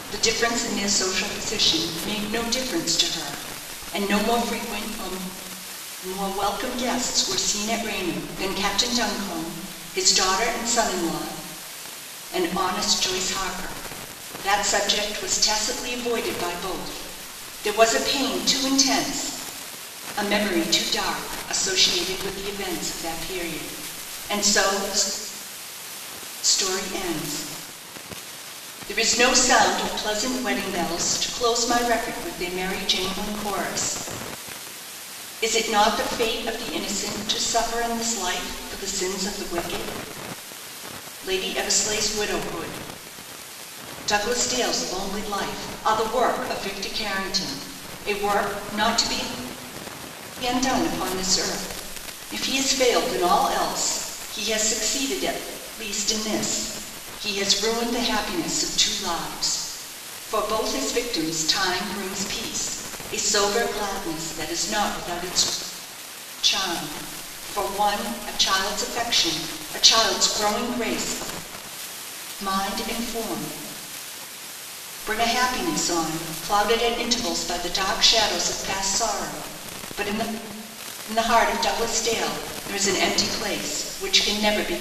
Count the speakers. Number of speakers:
one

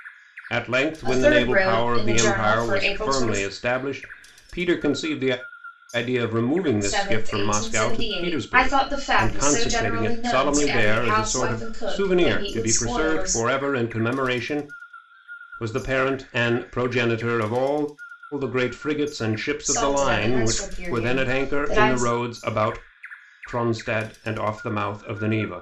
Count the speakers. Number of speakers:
two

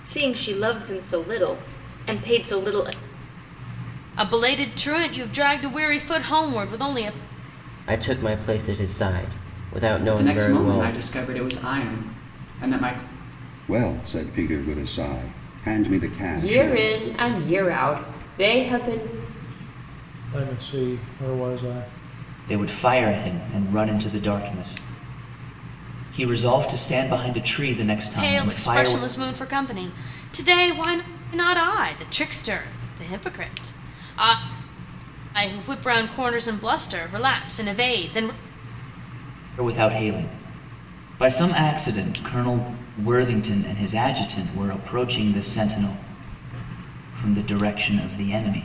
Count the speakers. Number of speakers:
eight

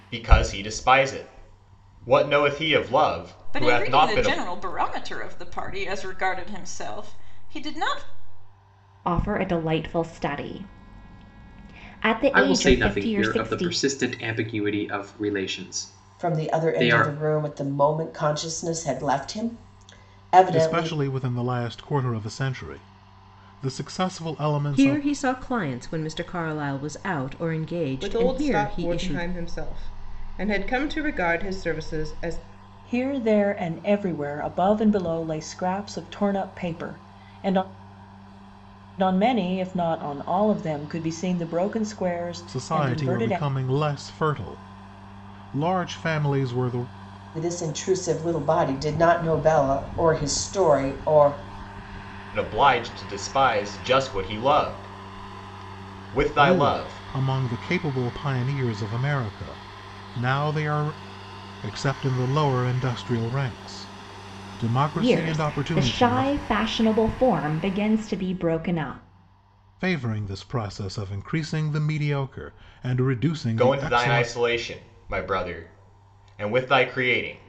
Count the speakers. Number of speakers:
nine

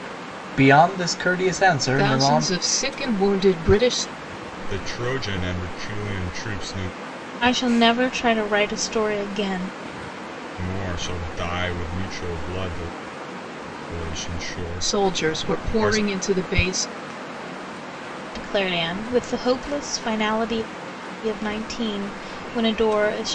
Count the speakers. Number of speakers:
four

